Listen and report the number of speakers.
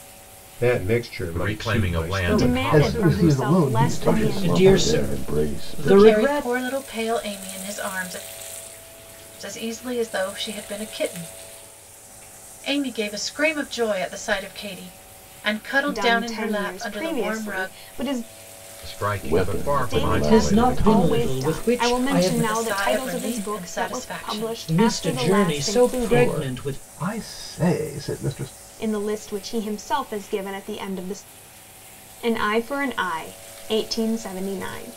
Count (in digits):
7